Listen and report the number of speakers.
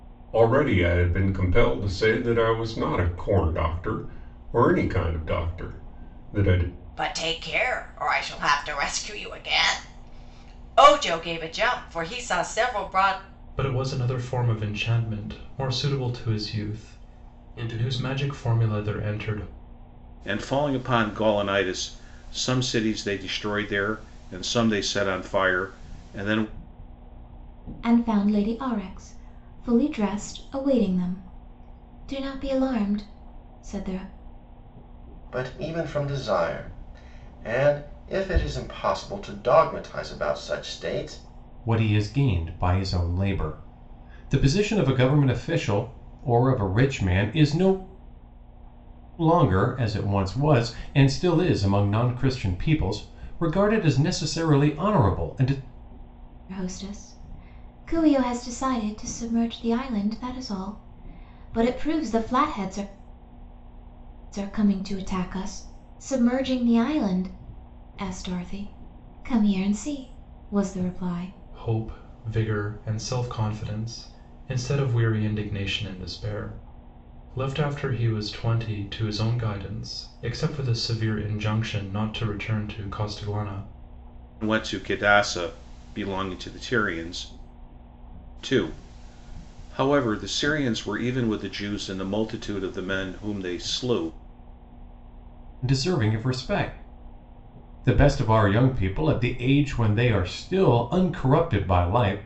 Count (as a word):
seven